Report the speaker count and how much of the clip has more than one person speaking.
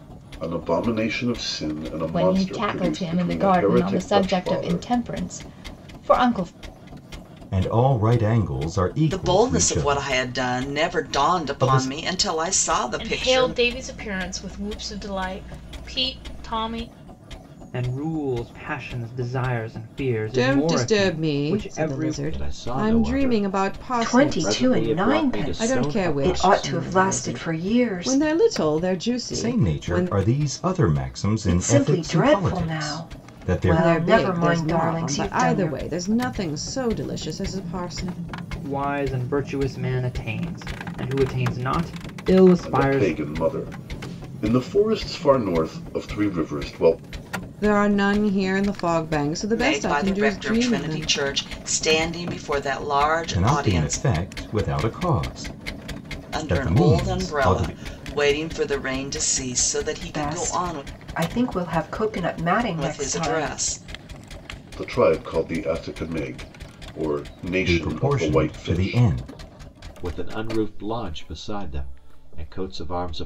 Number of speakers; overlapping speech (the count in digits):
9, about 36%